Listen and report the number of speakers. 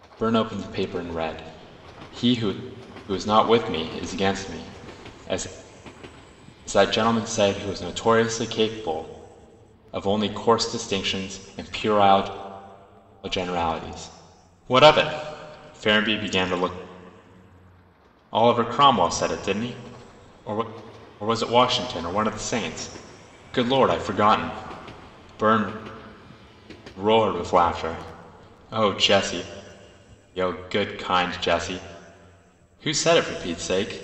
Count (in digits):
1